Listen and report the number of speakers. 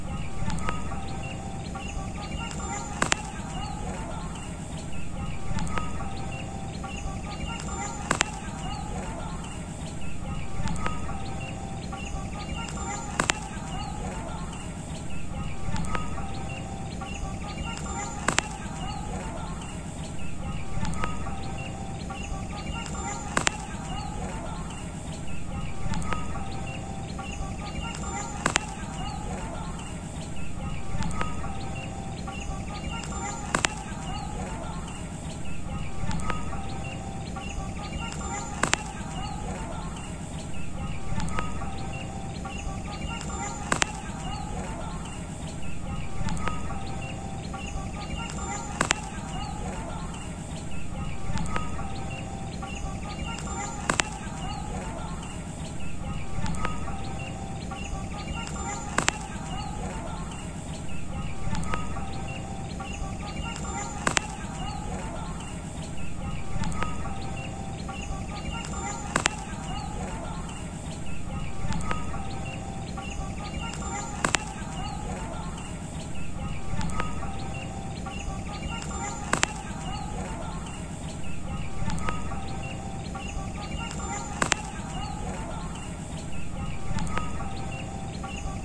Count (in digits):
0